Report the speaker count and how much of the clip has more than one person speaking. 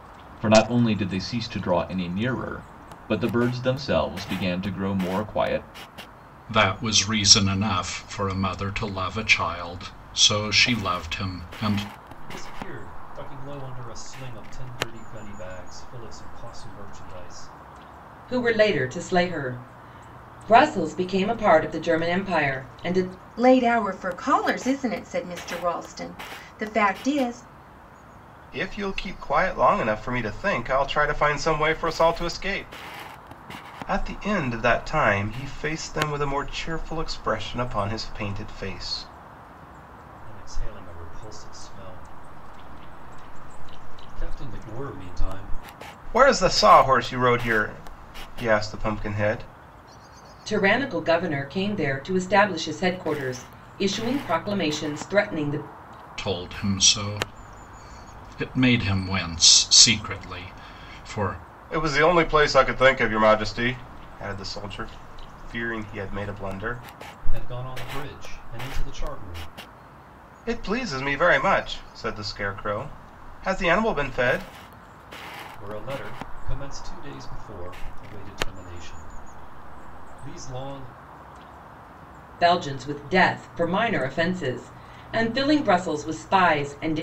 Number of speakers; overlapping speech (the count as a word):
six, no overlap